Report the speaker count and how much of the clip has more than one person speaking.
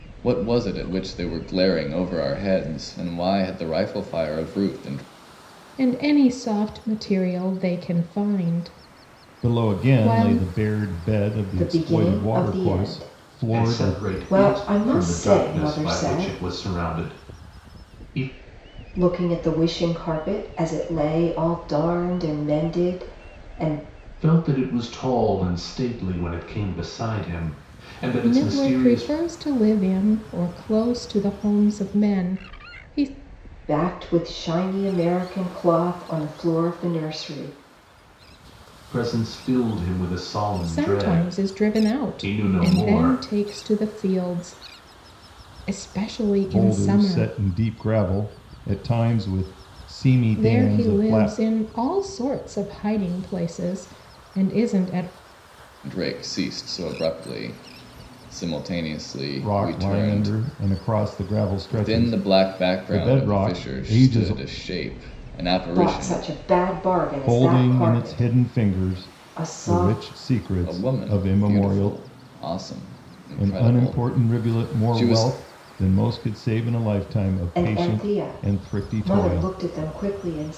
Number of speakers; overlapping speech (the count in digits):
5, about 29%